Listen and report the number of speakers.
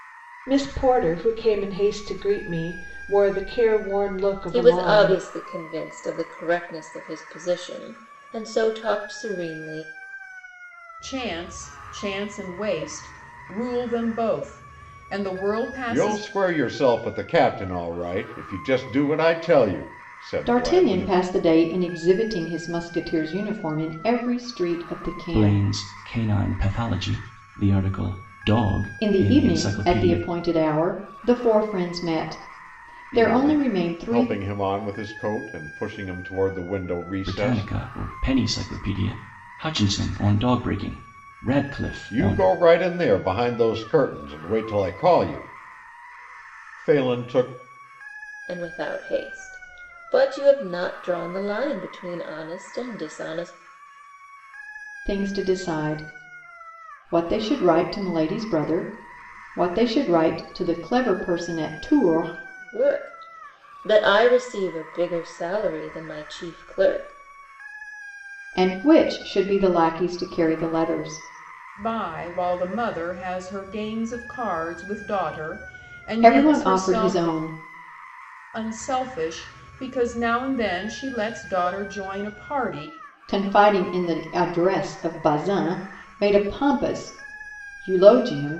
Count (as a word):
six